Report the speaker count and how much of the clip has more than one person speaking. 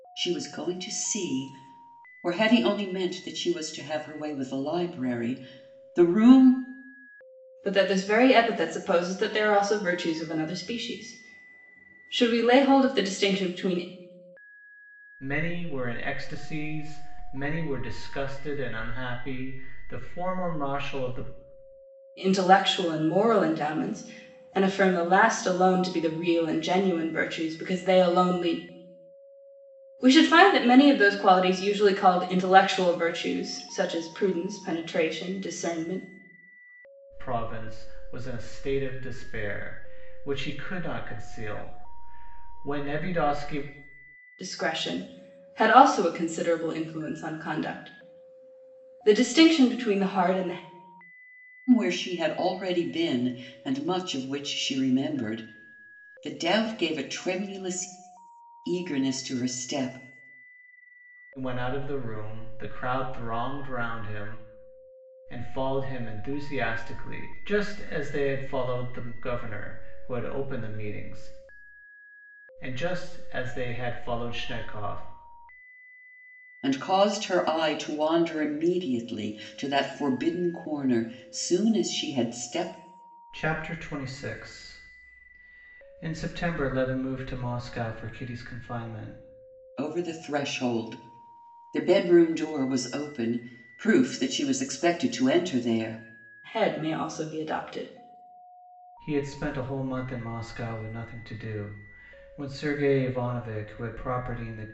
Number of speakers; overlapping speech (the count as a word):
three, no overlap